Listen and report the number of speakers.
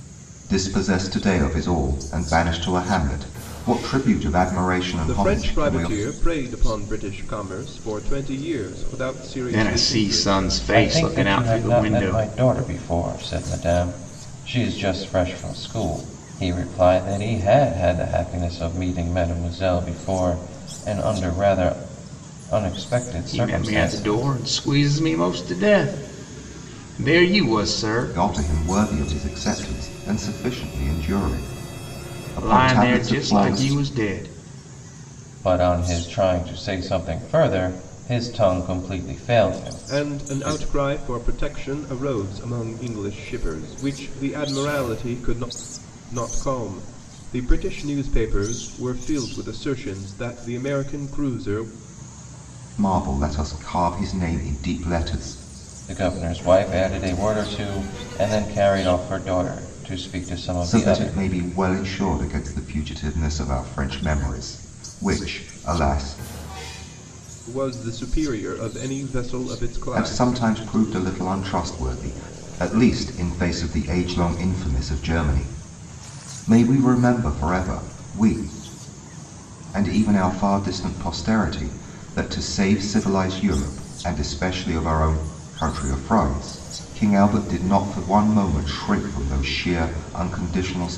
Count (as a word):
four